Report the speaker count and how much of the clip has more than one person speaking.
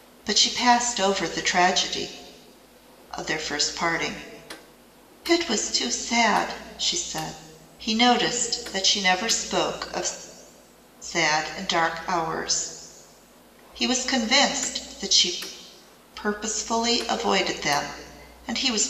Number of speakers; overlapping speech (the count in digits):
1, no overlap